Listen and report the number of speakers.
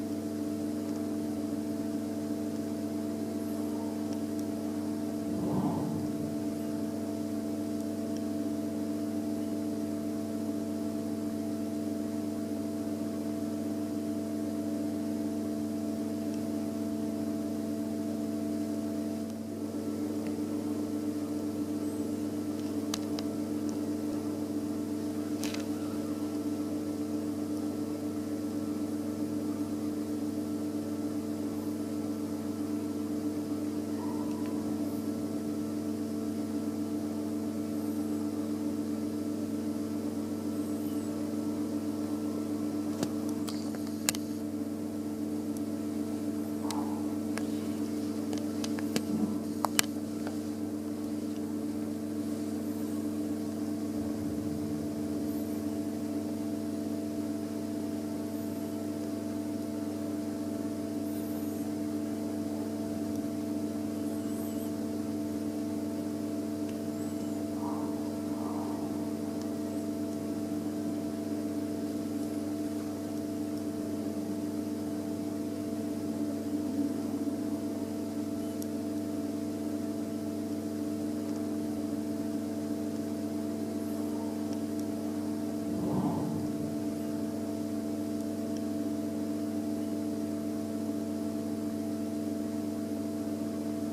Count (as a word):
zero